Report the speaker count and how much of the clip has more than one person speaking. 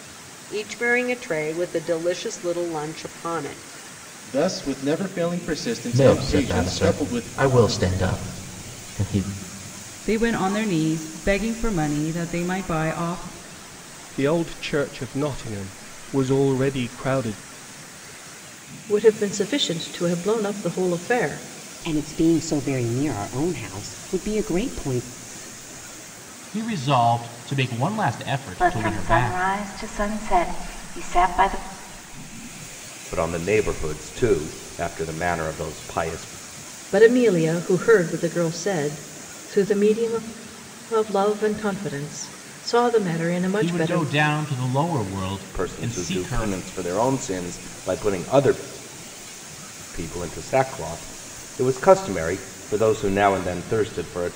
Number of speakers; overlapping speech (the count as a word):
ten, about 7%